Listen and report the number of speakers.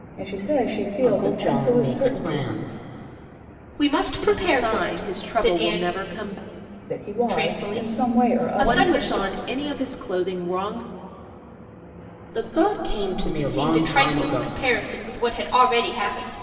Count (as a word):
four